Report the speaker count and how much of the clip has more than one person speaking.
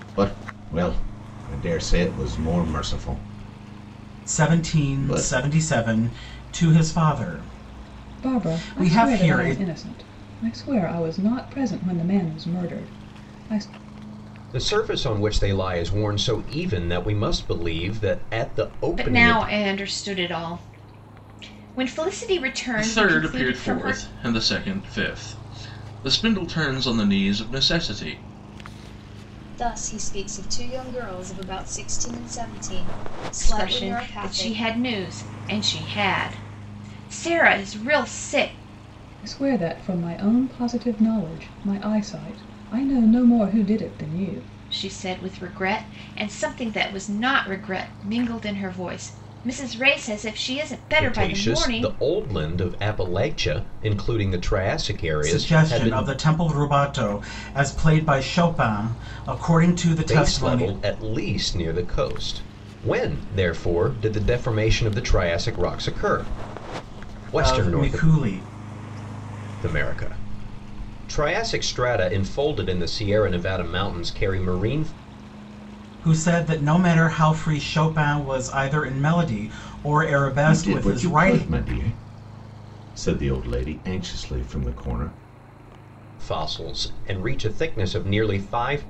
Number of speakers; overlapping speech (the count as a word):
seven, about 11%